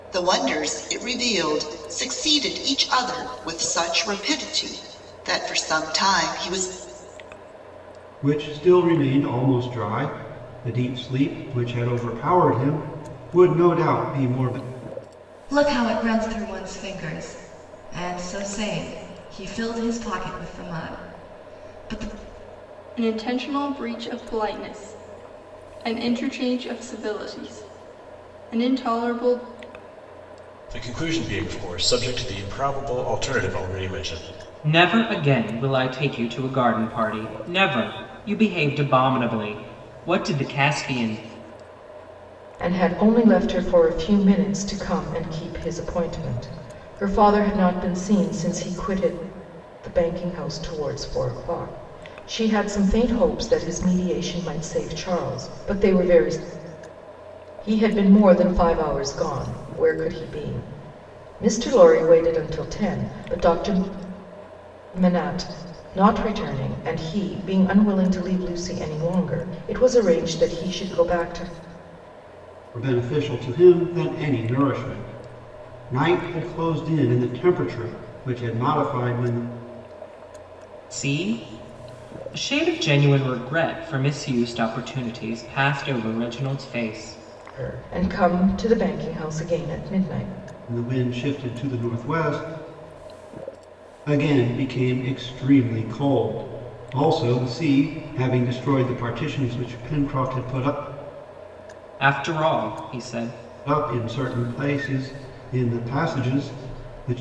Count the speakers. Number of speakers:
seven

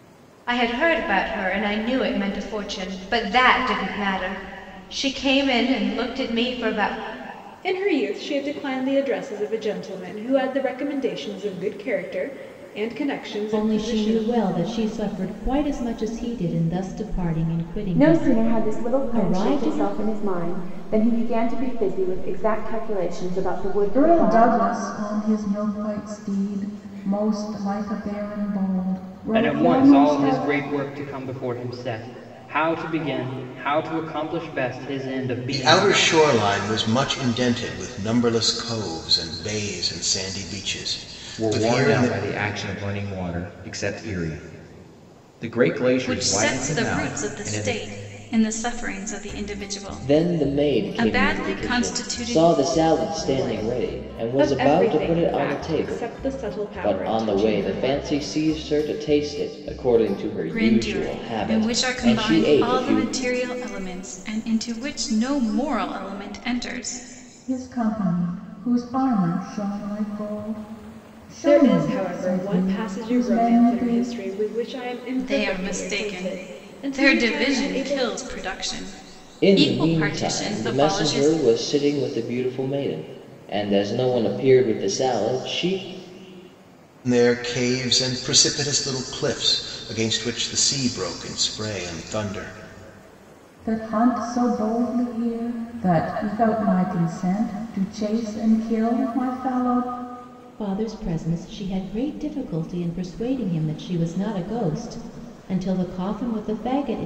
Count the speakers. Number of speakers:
ten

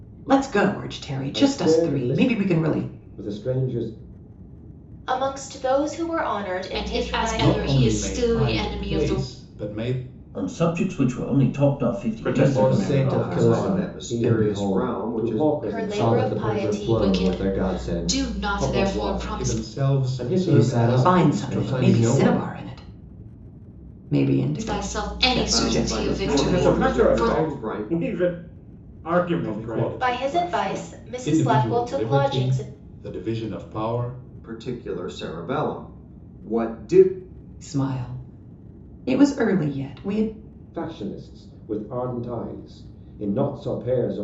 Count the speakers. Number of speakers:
nine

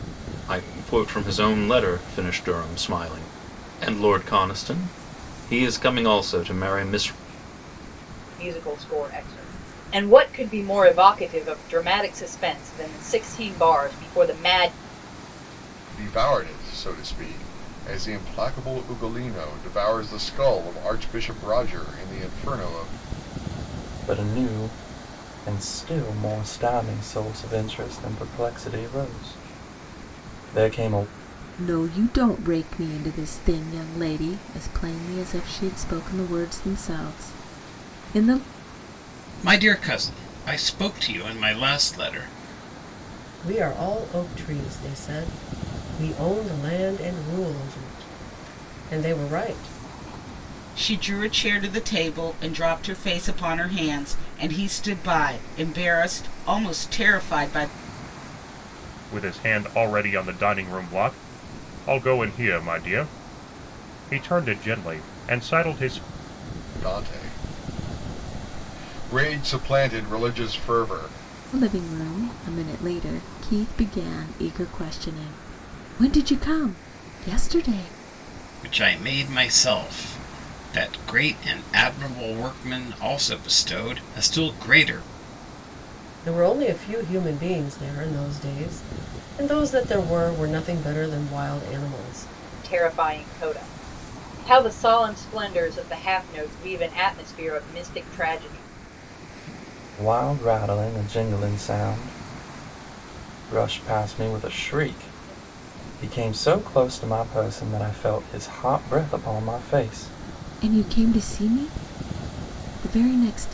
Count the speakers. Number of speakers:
nine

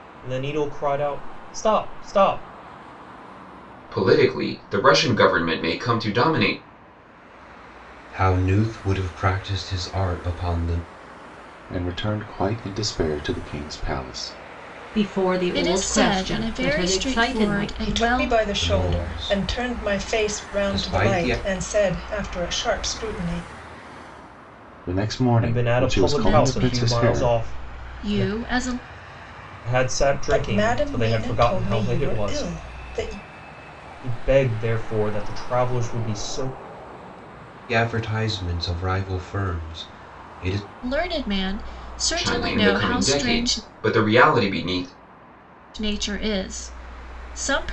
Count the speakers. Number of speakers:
seven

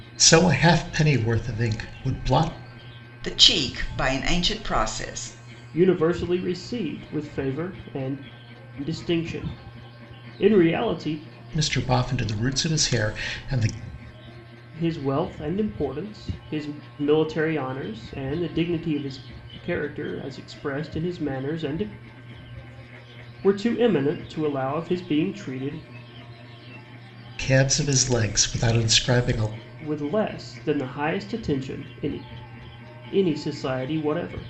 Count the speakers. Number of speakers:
three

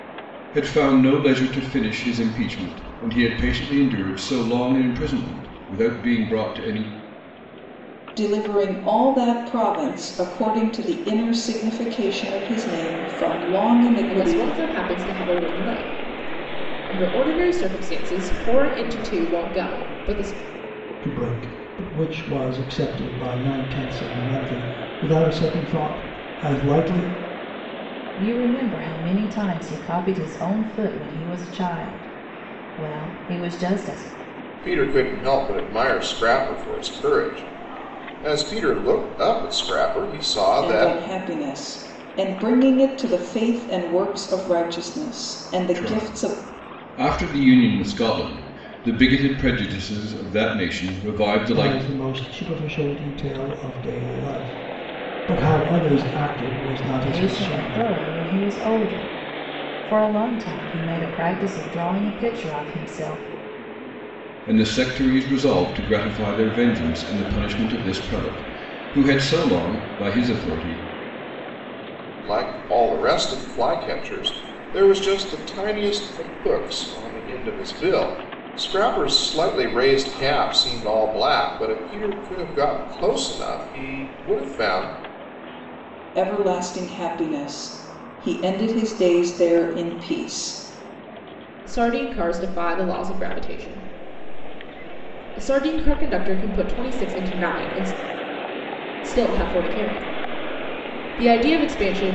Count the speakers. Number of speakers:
six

